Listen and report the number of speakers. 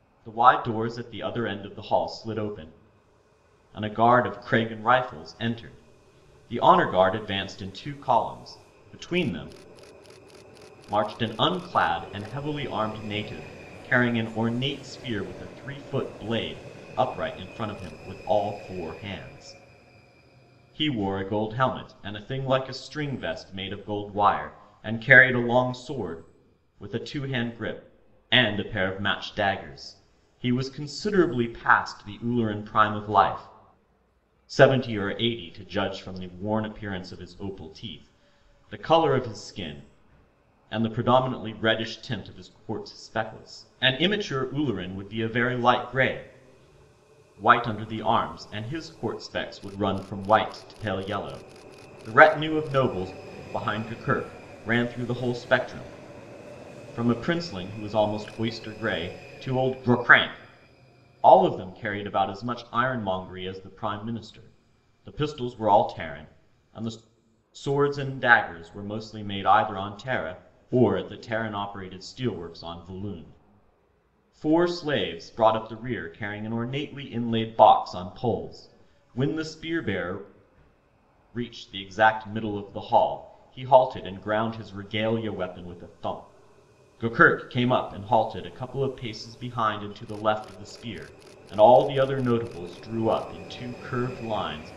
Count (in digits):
1